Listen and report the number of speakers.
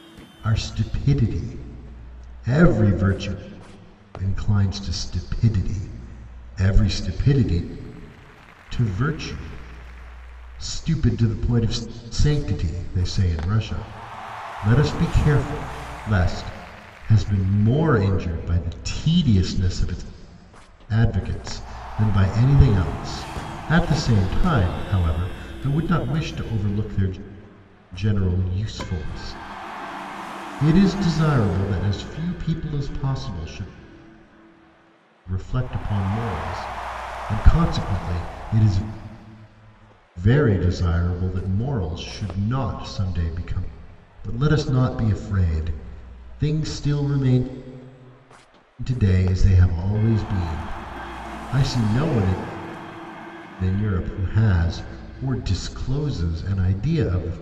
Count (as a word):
one